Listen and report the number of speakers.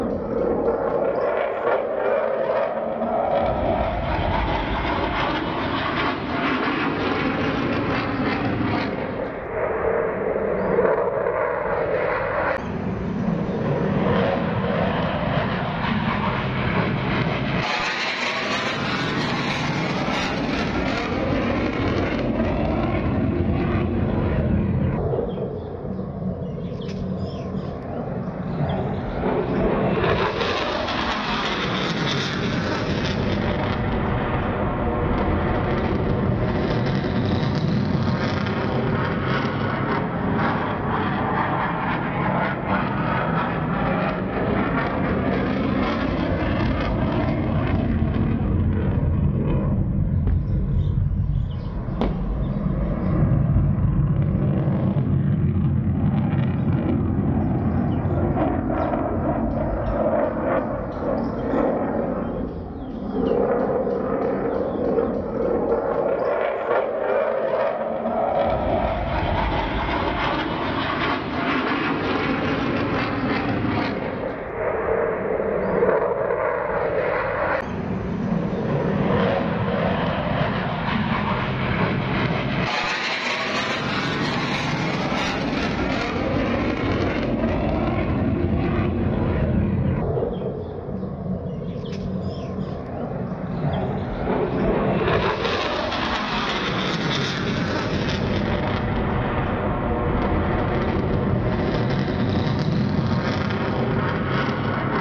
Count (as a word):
zero